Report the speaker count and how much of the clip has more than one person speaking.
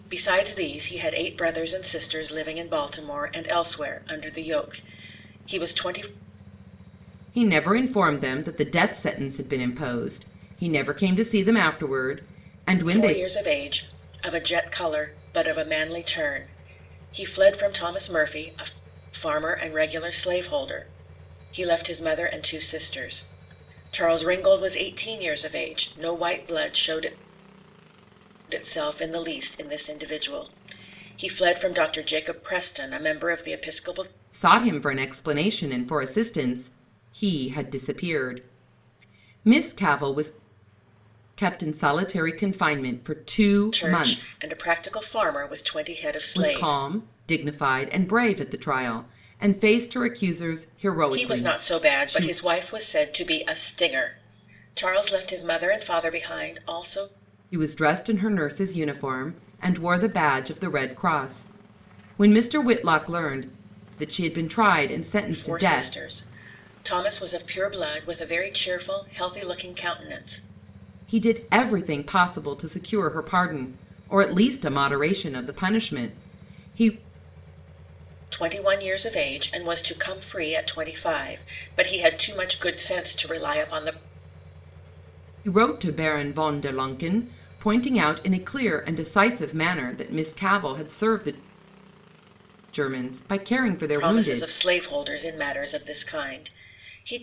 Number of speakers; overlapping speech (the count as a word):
two, about 4%